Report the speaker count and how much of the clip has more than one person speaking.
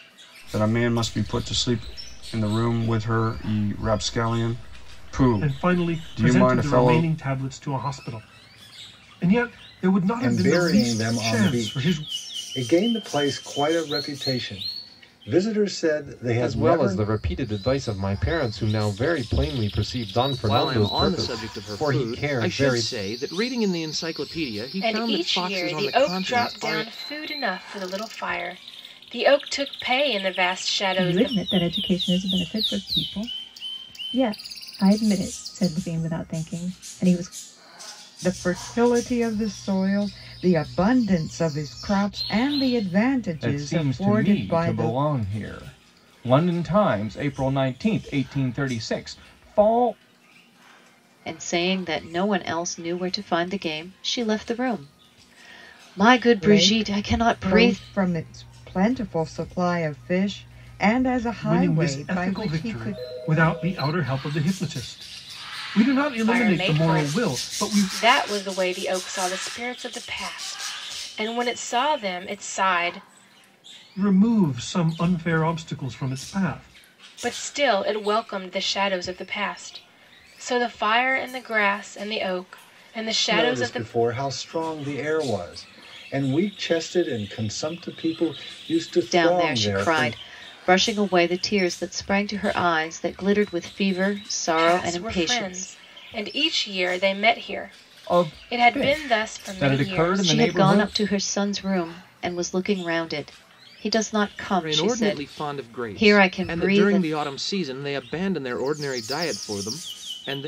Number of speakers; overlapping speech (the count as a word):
ten, about 22%